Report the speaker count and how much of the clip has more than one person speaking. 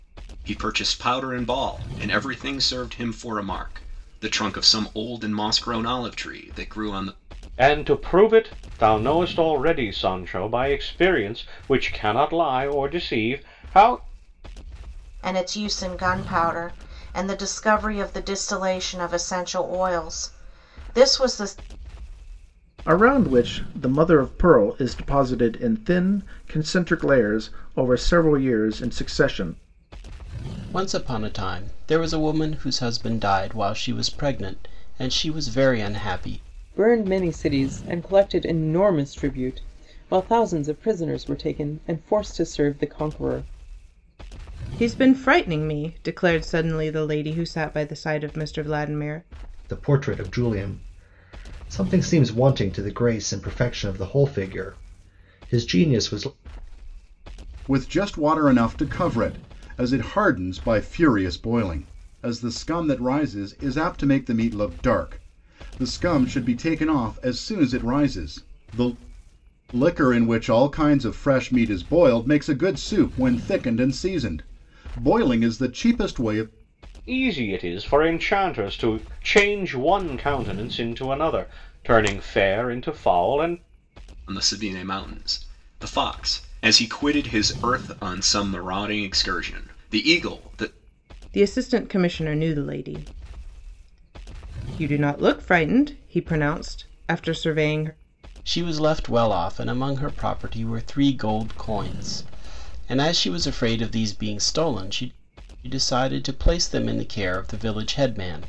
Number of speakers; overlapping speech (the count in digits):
9, no overlap